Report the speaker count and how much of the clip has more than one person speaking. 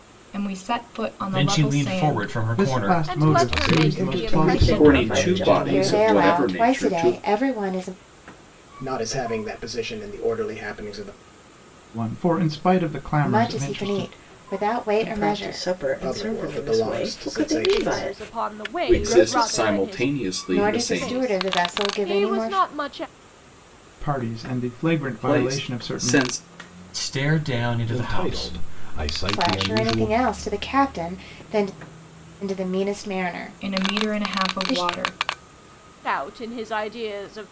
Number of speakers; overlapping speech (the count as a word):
nine, about 47%